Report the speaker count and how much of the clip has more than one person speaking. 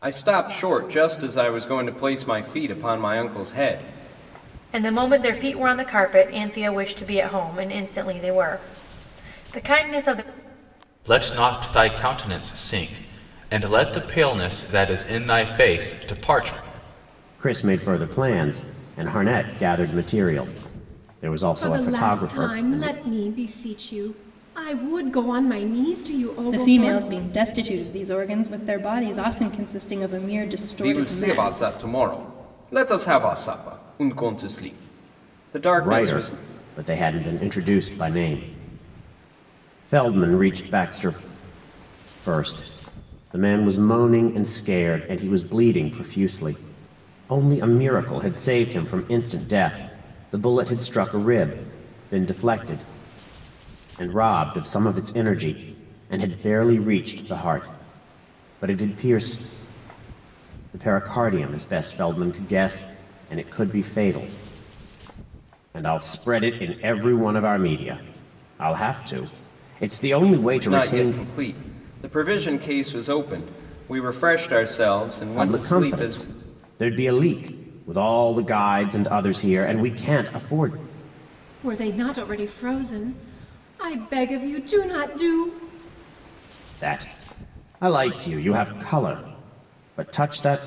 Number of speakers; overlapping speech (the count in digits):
6, about 6%